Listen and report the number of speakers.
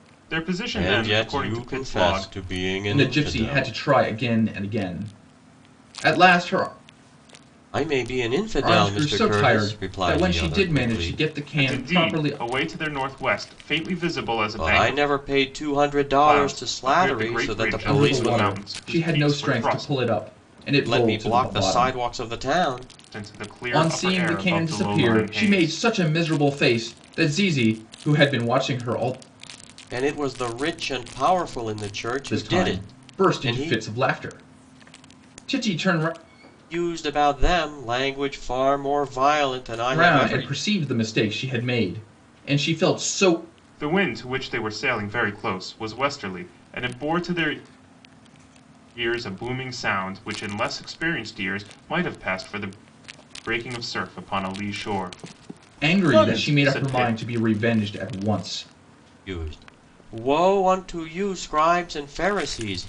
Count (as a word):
three